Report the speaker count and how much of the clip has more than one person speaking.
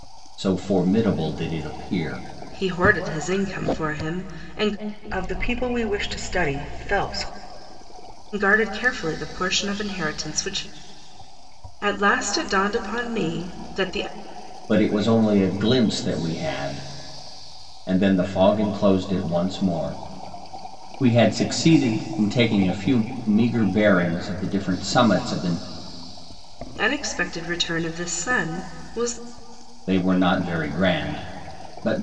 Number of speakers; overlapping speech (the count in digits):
3, no overlap